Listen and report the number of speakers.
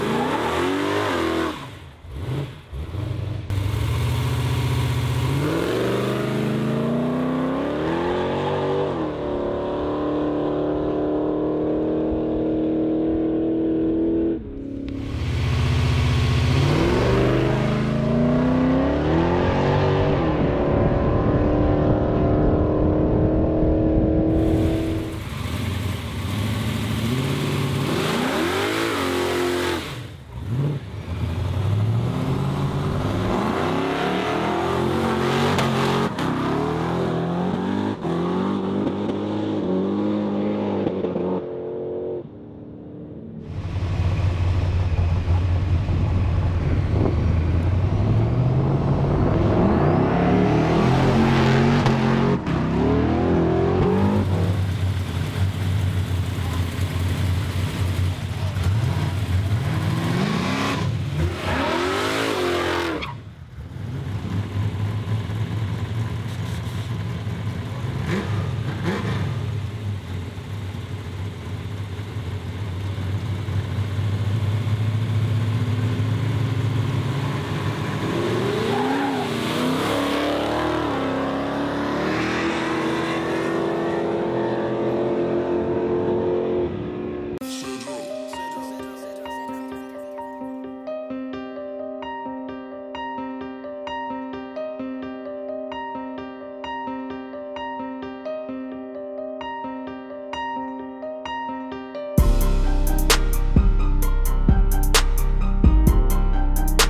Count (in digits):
0